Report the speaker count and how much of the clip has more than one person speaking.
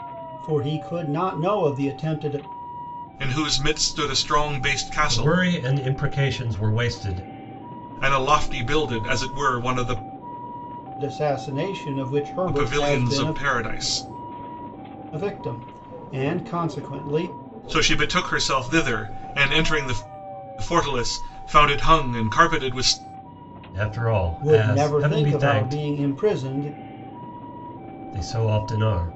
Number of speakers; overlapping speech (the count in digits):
3, about 9%